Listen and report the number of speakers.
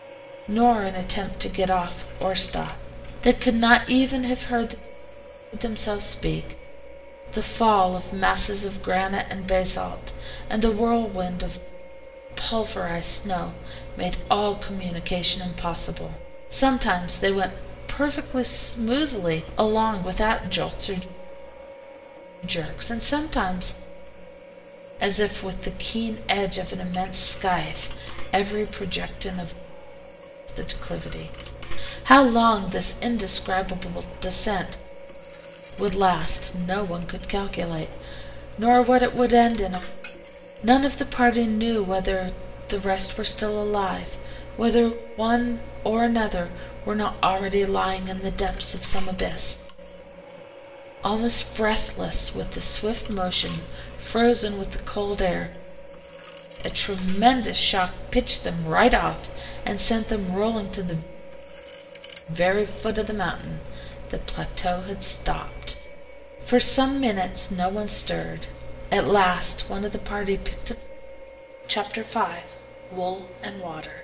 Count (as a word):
one